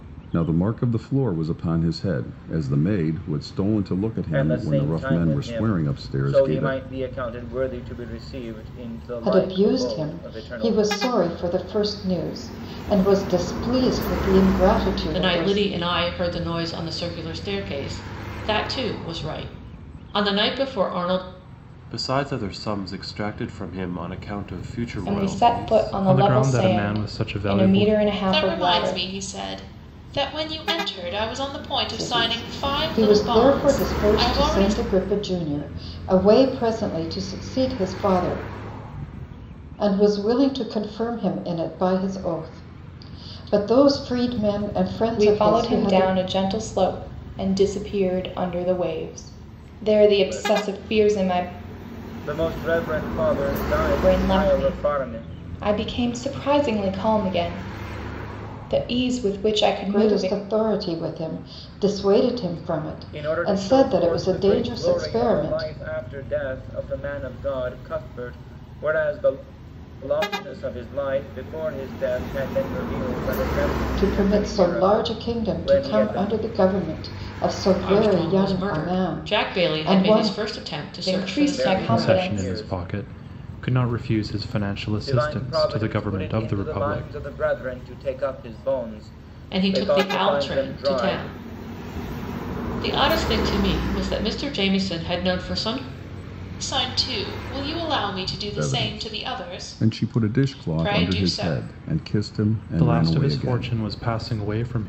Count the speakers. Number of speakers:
7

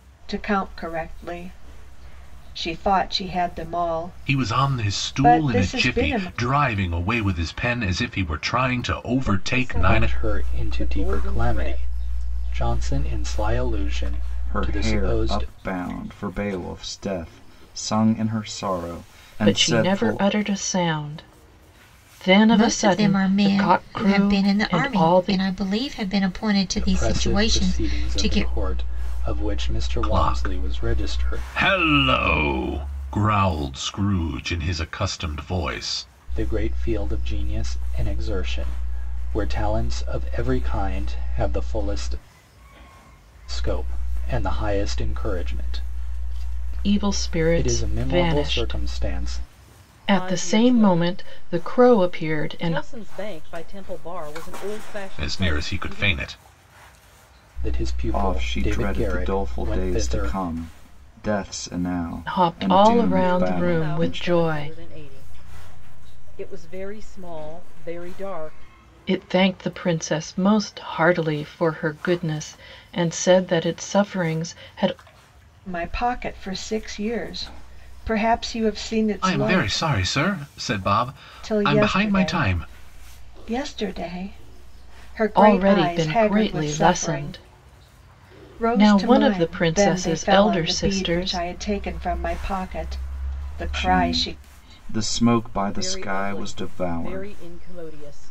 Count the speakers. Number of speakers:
7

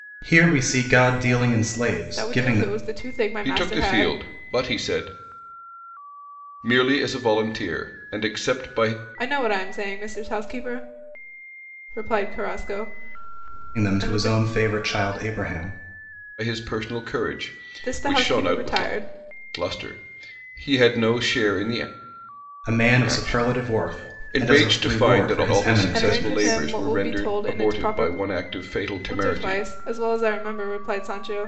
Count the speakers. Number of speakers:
3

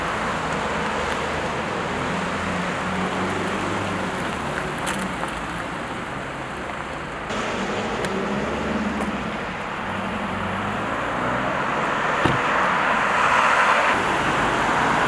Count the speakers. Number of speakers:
0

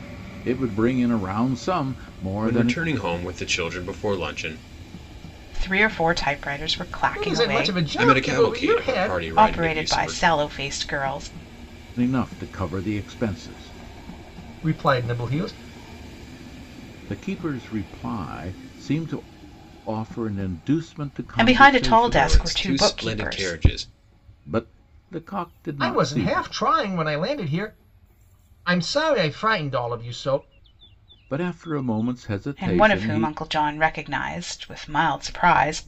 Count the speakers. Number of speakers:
4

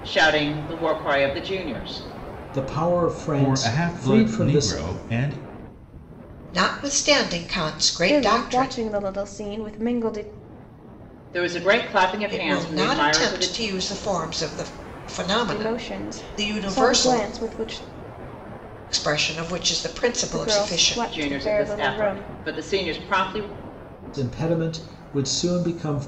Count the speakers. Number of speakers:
5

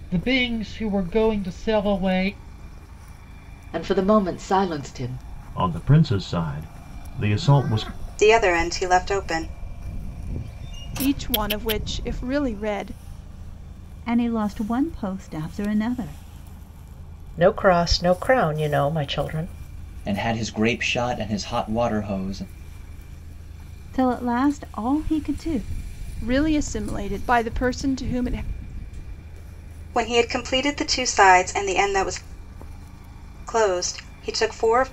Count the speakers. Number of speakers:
8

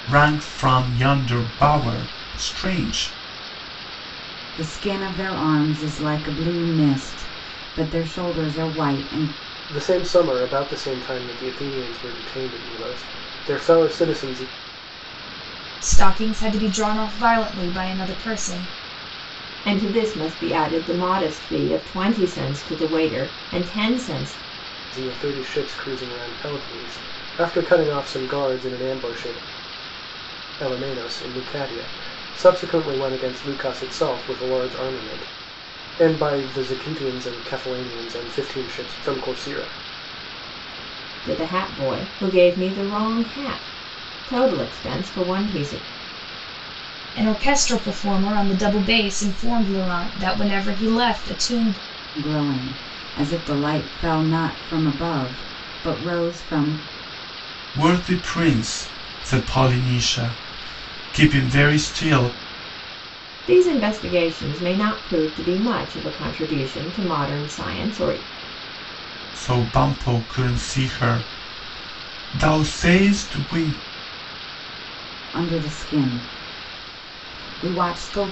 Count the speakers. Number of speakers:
5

